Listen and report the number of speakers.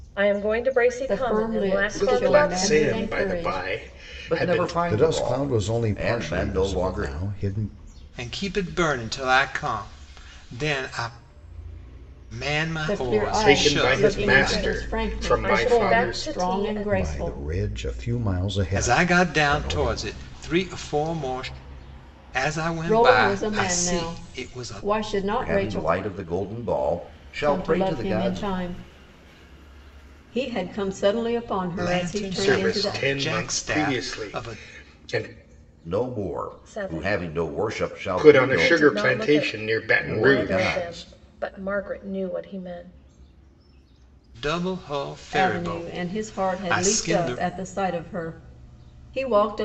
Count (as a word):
six